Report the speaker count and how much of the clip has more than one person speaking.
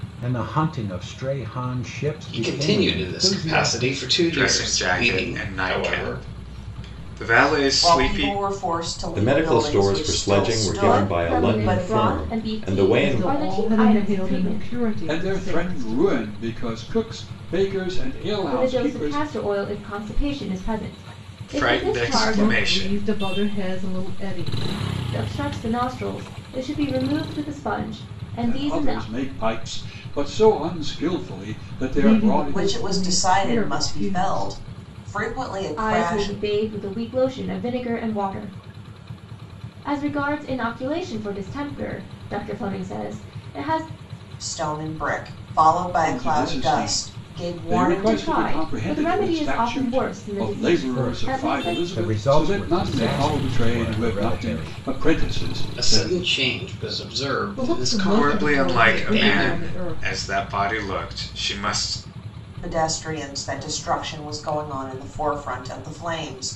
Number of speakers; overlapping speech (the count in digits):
8, about 44%